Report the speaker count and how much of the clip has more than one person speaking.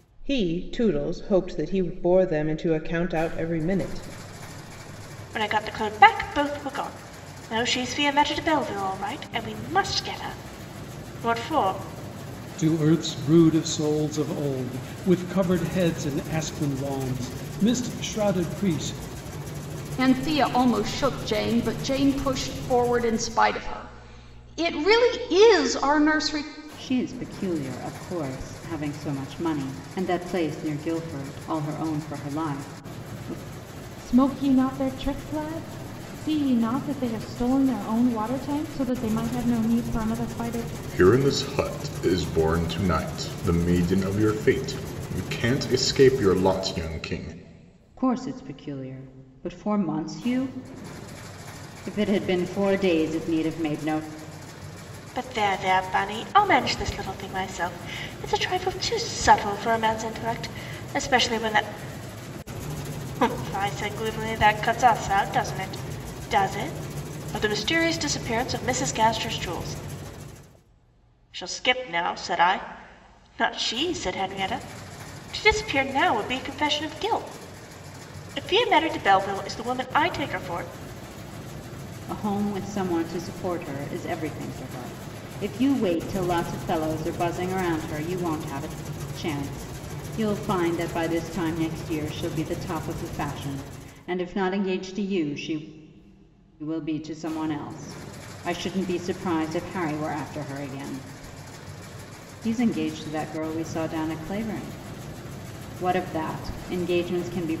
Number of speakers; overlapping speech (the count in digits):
7, no overlap